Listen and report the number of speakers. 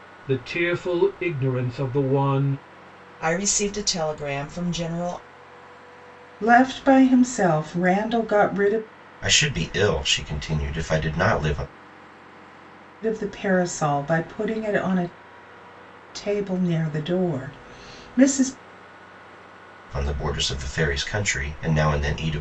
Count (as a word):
four